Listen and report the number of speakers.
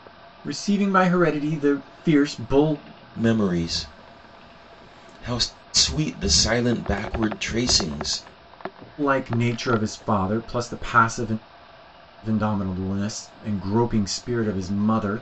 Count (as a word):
two